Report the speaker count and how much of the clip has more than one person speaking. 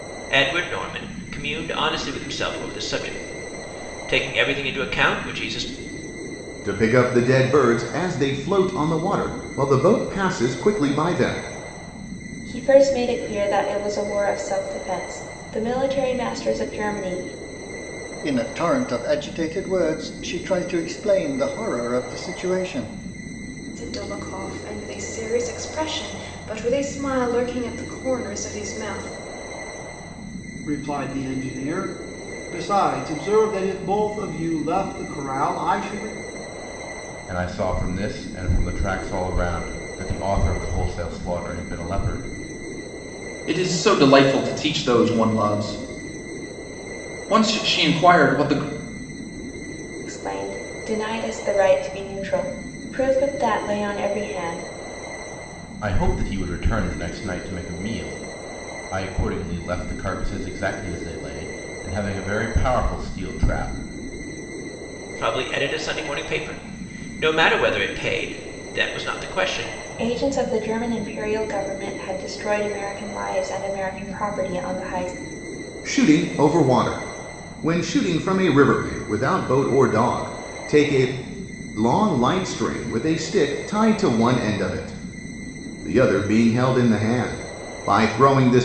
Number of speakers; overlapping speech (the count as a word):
eight, no overlap